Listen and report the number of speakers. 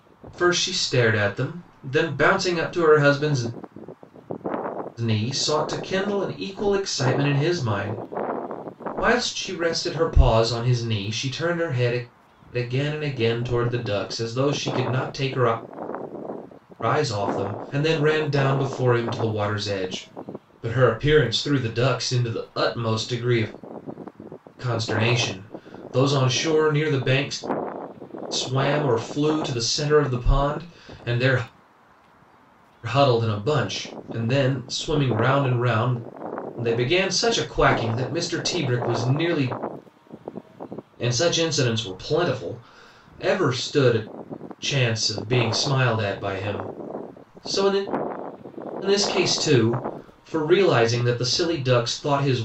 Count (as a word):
one